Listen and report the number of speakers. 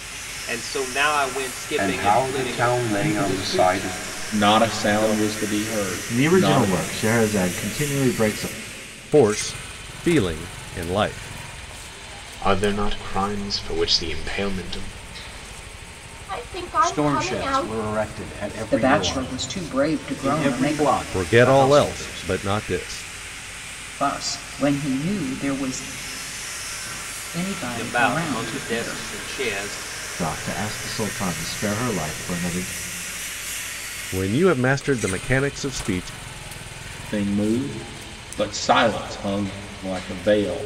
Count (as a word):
ten